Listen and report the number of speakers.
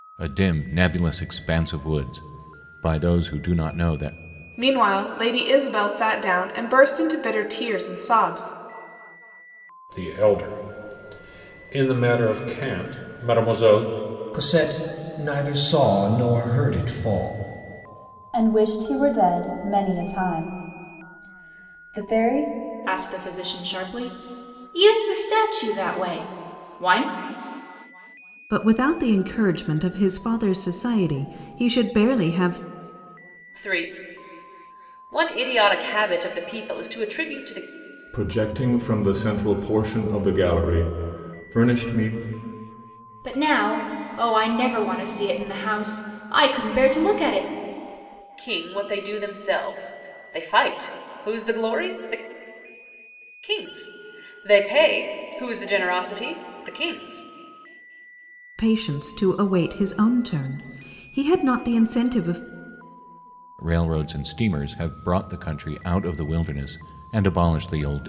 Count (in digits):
9